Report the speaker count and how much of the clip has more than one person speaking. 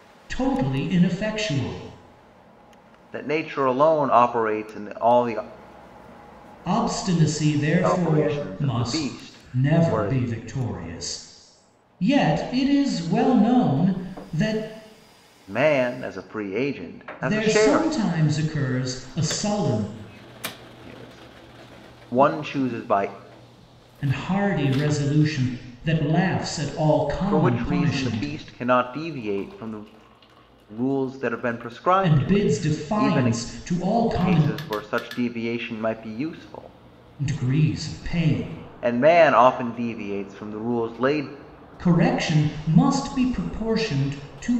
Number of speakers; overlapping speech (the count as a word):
two, about 13%